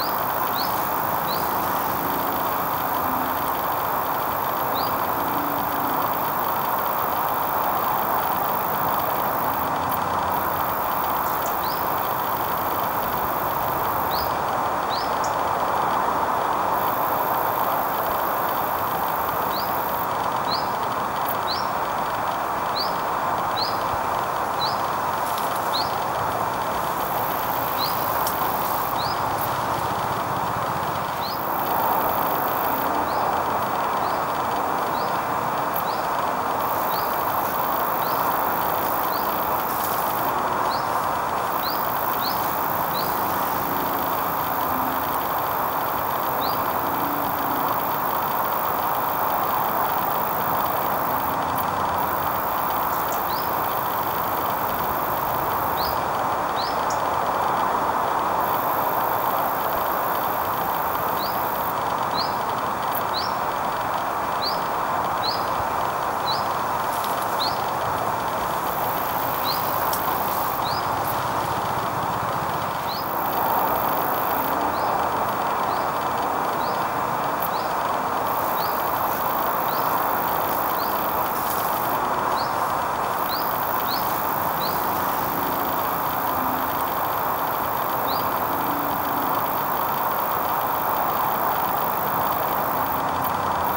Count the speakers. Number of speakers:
zero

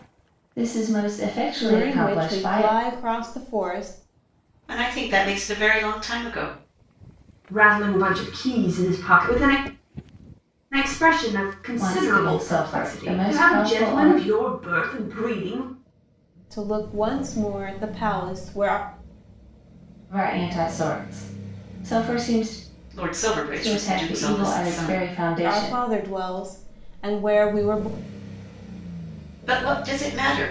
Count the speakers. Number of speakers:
four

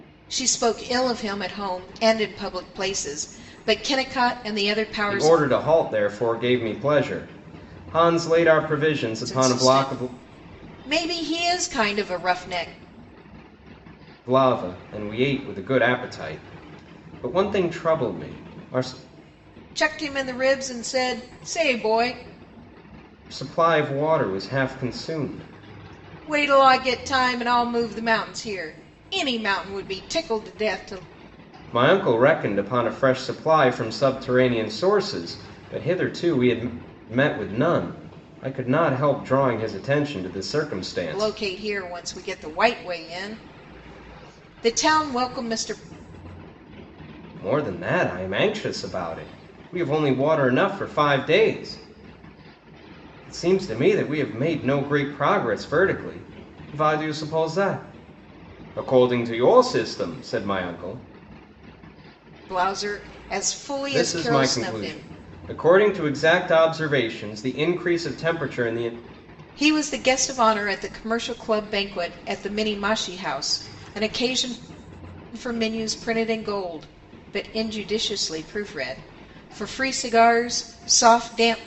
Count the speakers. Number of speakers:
two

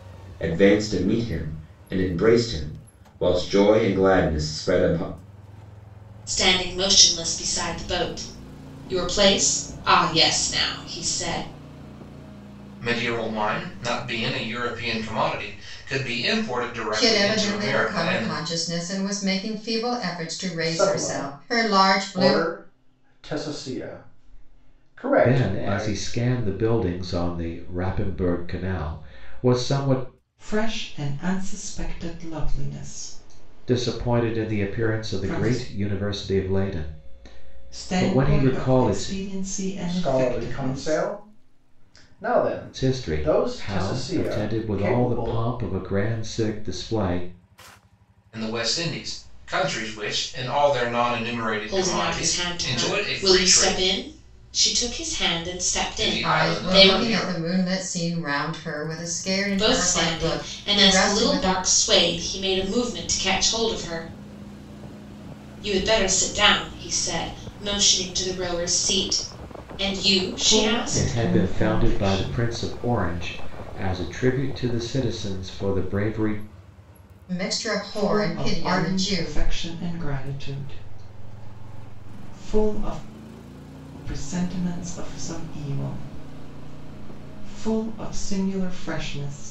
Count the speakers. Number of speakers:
seven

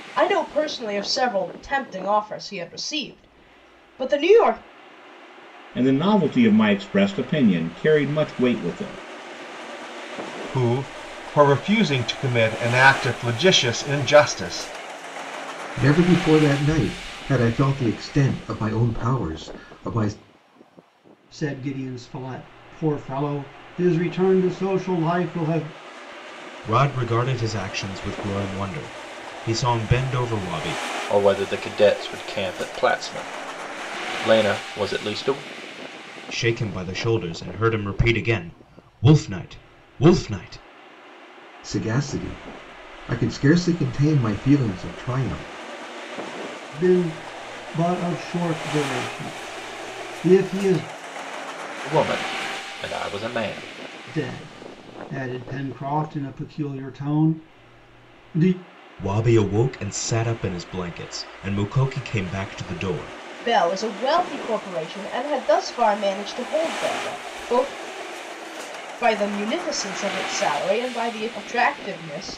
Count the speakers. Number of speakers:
seven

